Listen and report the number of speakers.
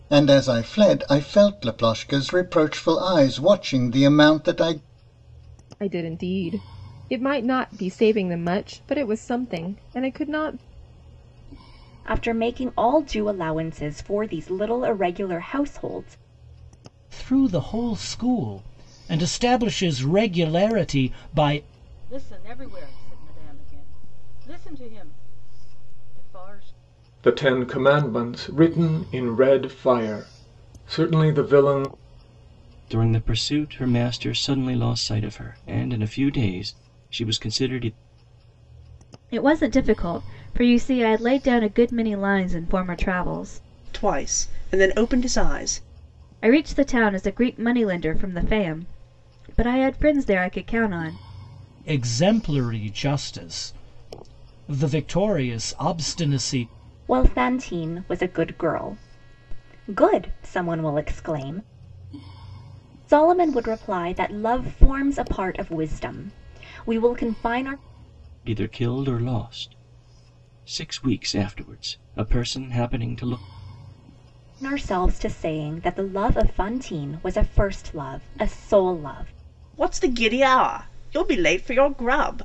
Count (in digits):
9